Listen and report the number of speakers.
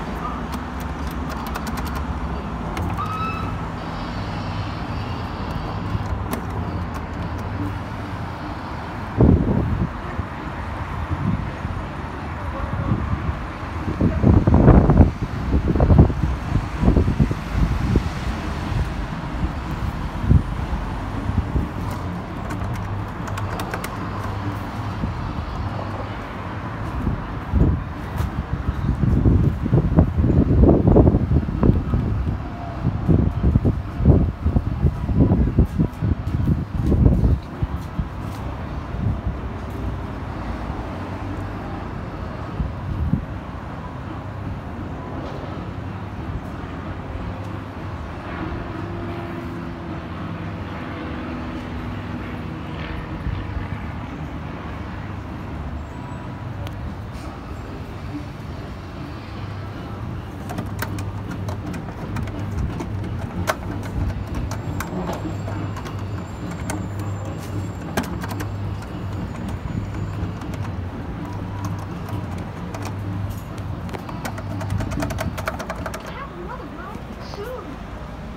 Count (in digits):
0